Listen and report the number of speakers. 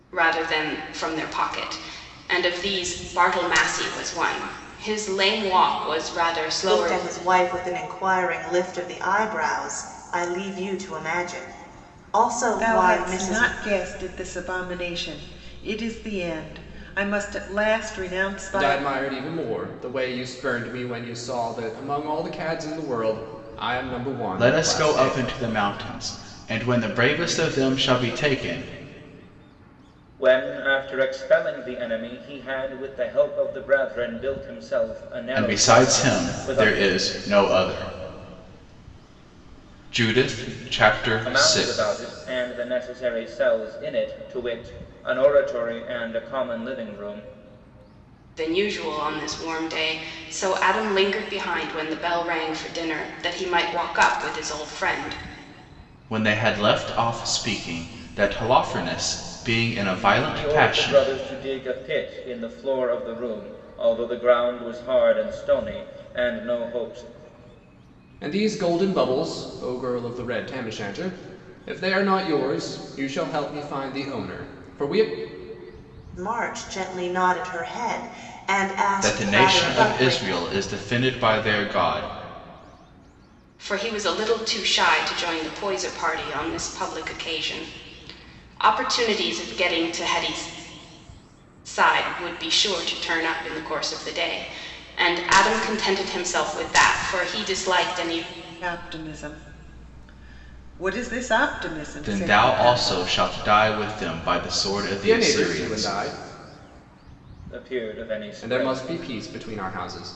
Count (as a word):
six